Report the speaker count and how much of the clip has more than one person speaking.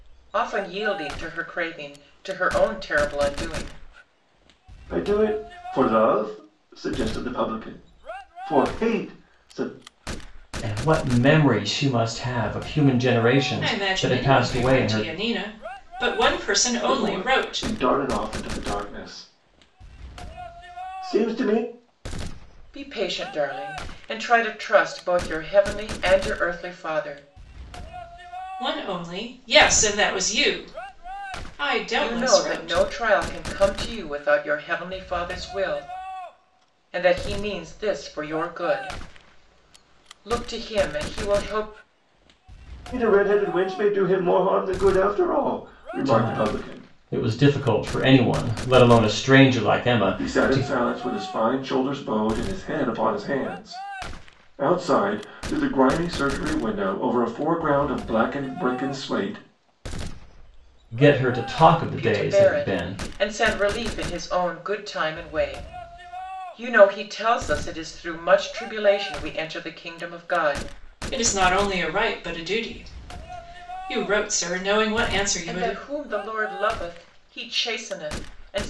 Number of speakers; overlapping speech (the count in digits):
4, about 8%